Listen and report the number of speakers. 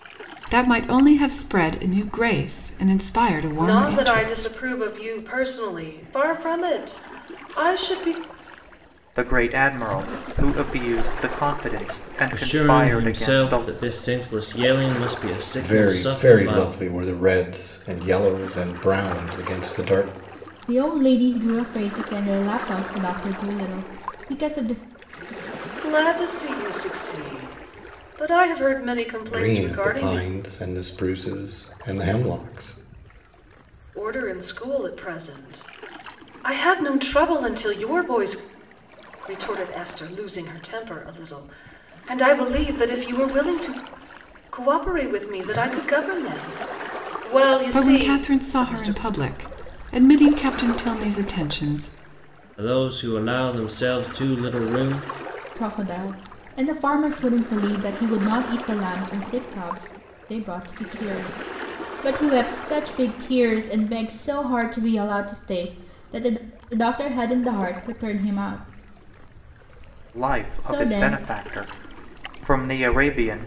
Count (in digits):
6